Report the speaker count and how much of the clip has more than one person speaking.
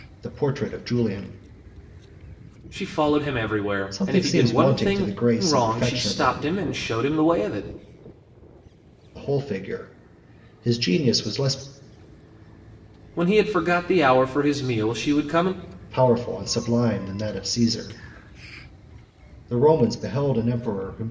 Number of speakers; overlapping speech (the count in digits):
2, about 10%